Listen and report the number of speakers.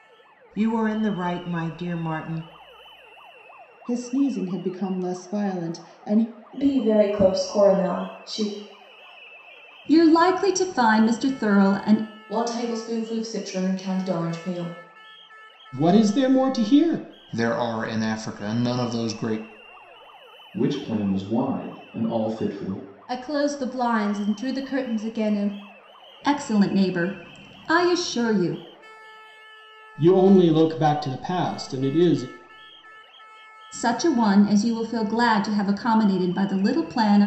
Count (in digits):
9